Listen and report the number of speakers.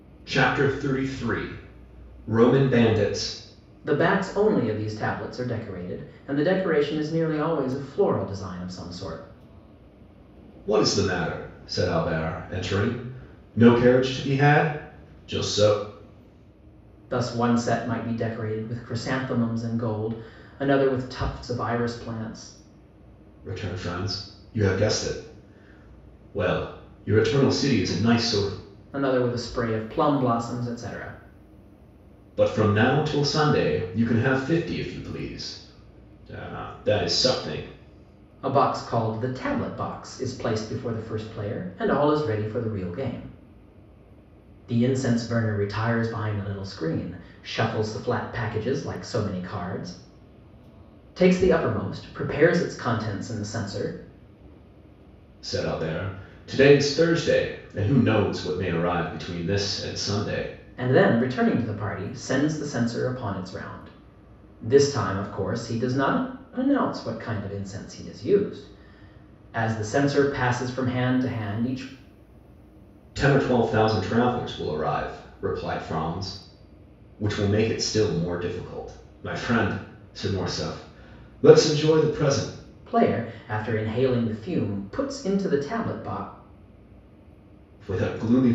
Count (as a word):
two